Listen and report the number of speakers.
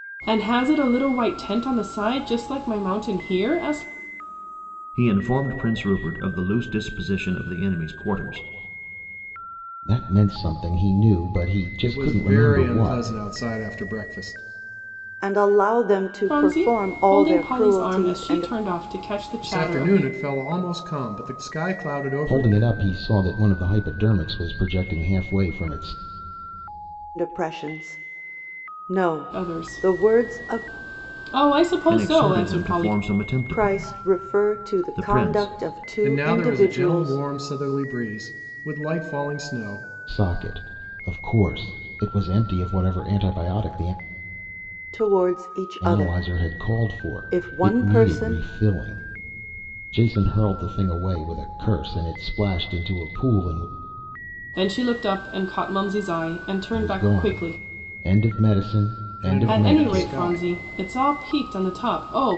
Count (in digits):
5